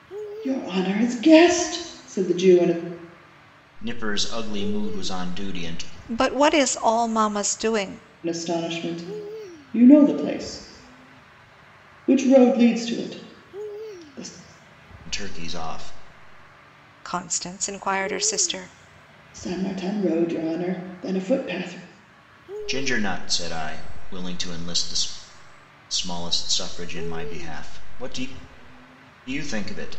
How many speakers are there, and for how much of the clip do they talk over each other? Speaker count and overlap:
three, no overlap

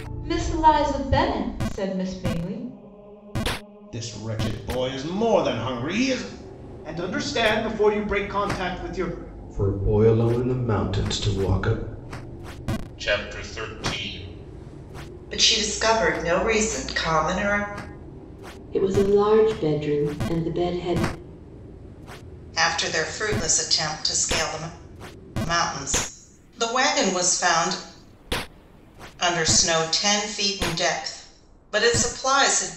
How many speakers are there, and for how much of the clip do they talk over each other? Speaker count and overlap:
eight, no overlap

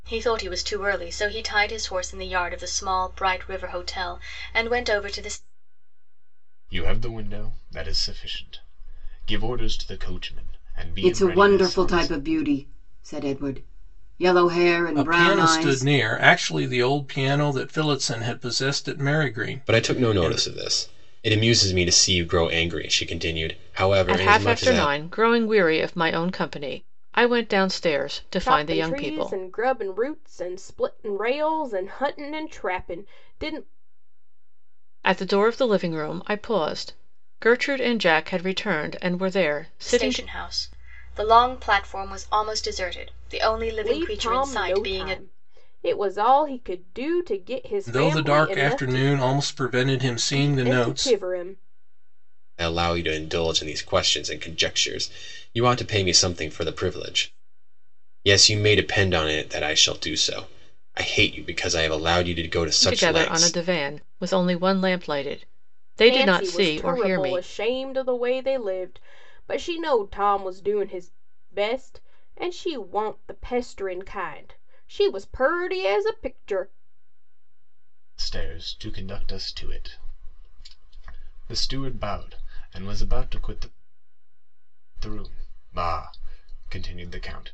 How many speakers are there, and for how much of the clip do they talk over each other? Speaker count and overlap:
seven, about 12%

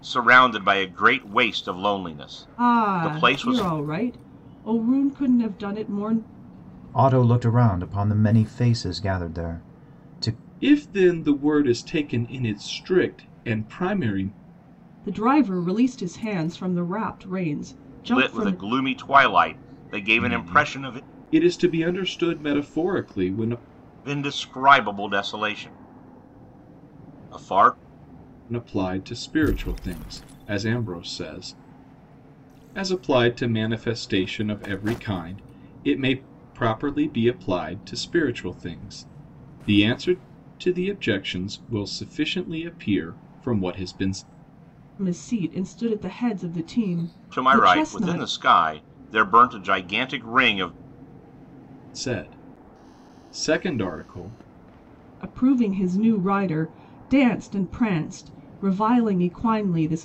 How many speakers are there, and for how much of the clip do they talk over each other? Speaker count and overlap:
four, about 6%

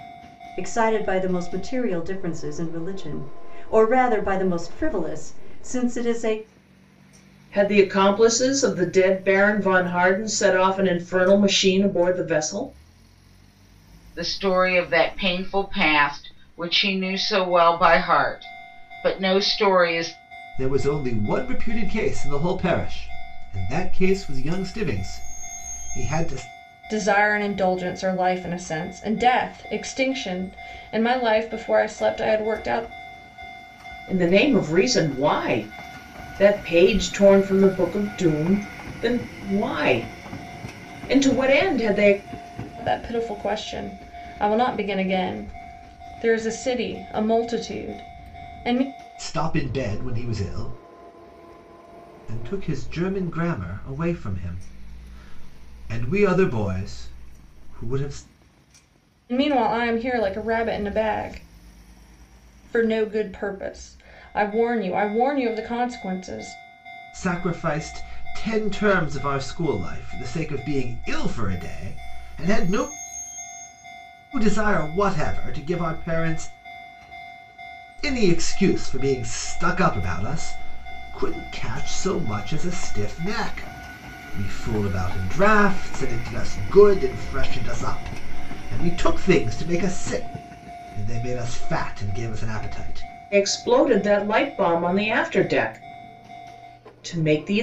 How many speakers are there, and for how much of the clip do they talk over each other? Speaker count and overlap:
five, no overlap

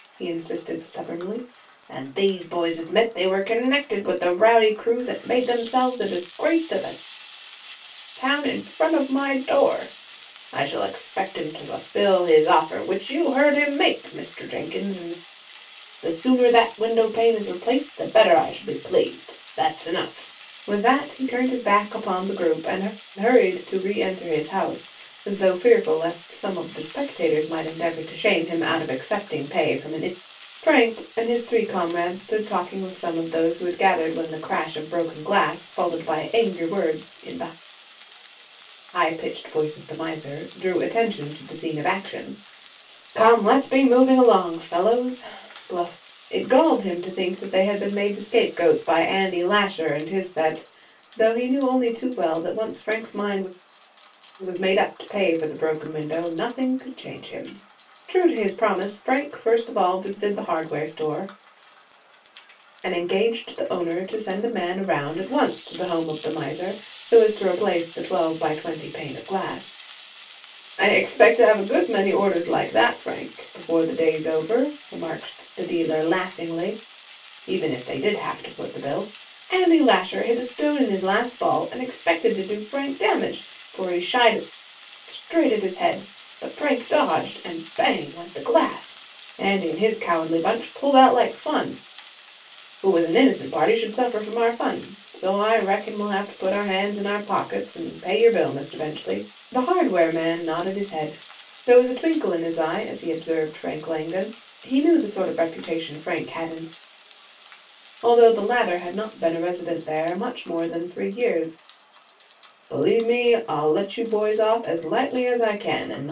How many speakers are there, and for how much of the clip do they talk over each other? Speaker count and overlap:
one, no overlap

